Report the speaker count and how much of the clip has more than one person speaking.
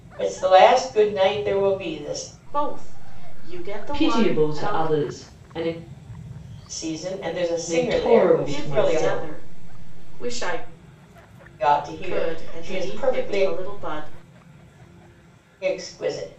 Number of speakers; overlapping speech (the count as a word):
three, about 26%